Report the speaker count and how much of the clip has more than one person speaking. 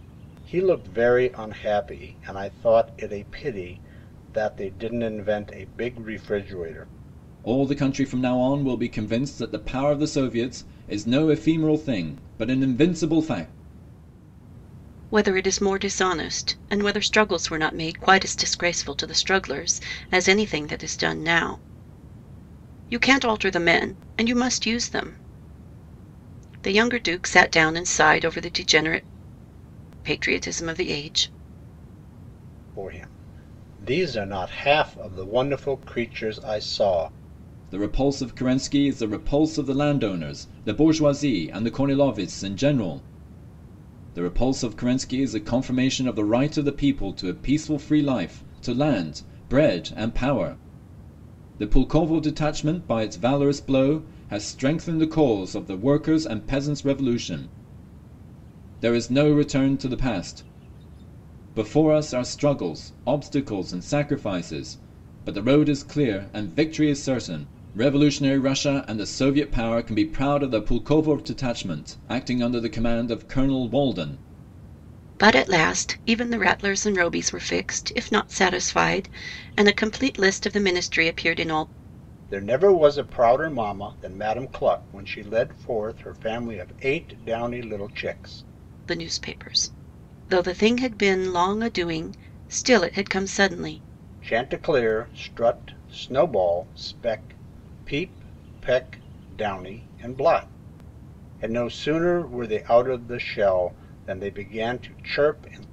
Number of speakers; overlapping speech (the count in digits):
3, no overlap